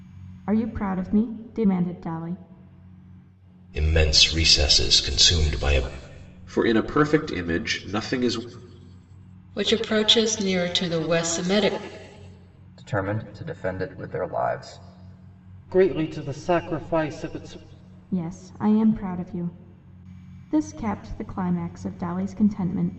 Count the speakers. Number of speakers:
six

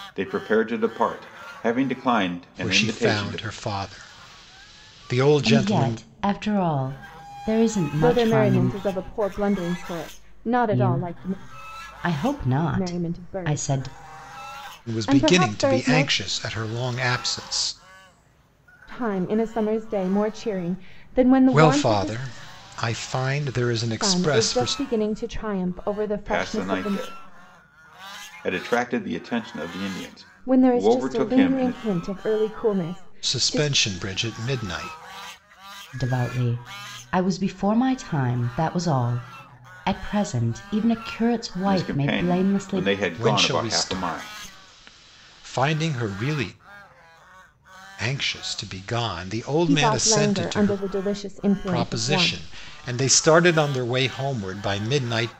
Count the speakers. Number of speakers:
four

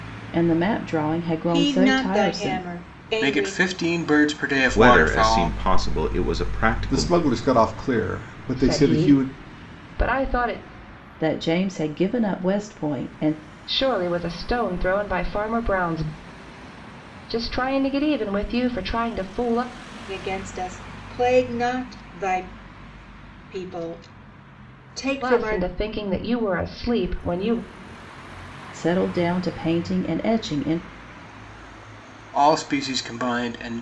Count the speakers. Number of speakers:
six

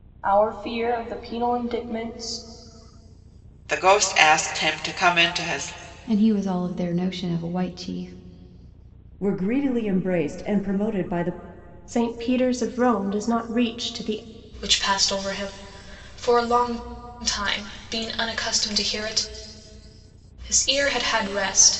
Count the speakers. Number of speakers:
six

